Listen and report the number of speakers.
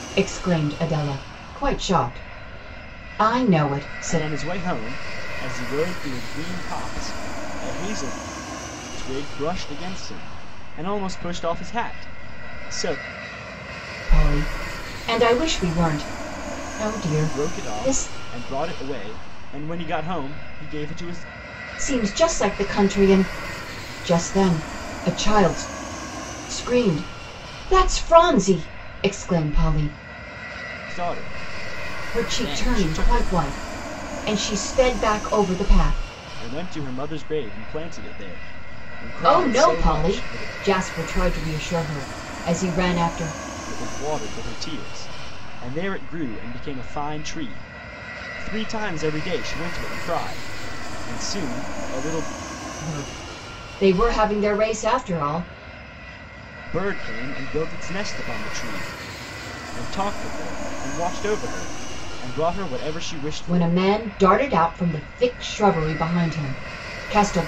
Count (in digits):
2